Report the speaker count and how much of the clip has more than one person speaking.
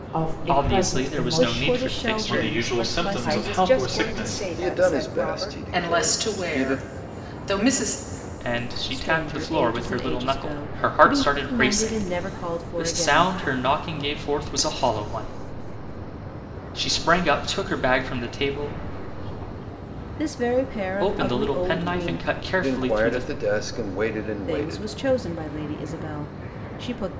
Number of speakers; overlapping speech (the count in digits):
7, about 47%